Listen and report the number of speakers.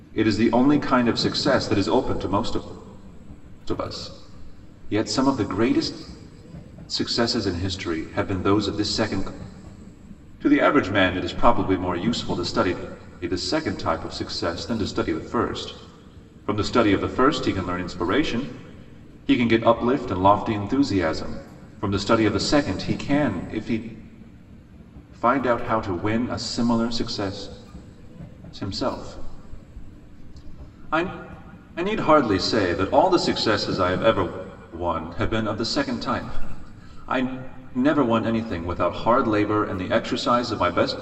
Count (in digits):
1